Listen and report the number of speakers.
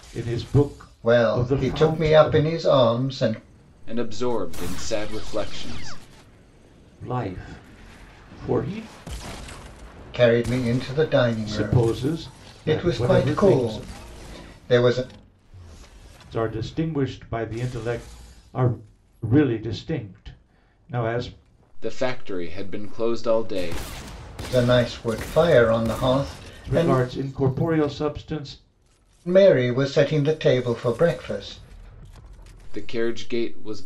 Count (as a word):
three